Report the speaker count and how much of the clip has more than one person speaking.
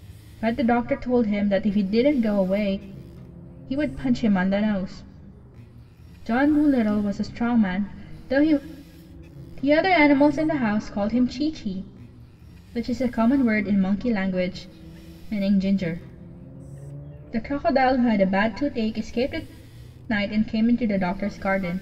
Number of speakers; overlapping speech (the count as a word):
one, no overlap